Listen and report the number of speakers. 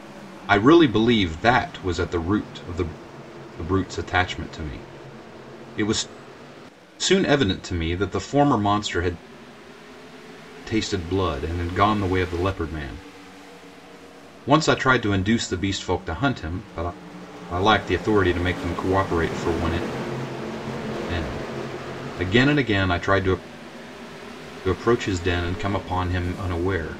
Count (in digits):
1